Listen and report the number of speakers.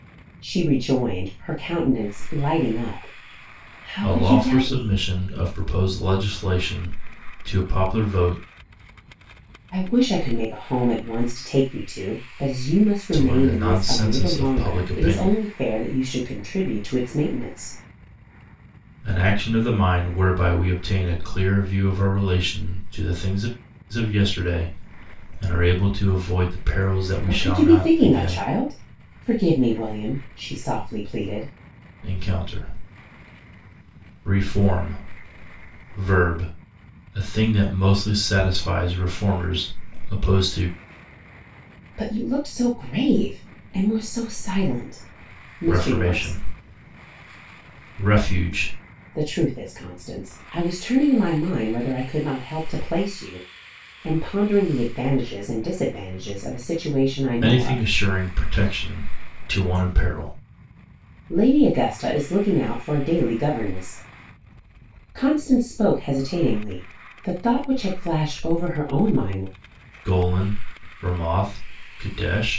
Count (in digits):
2